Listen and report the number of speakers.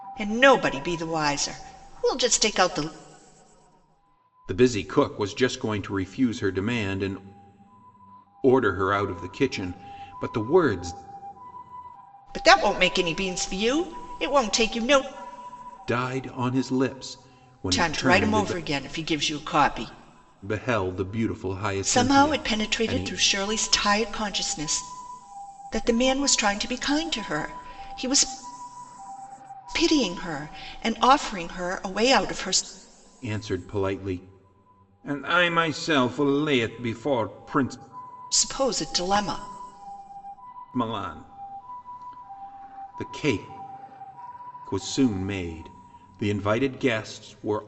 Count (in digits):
2